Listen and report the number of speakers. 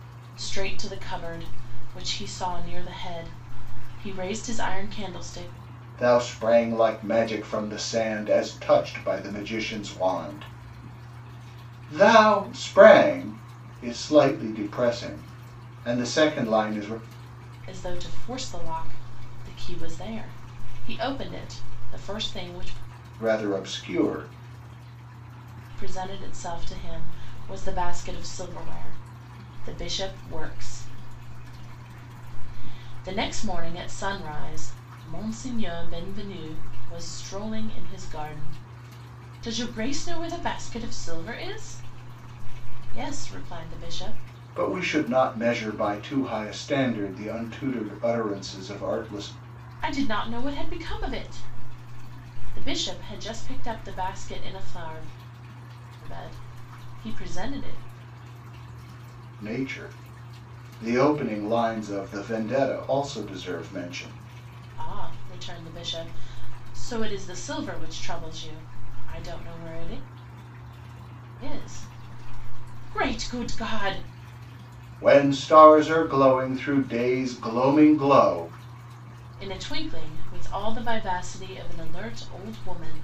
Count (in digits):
2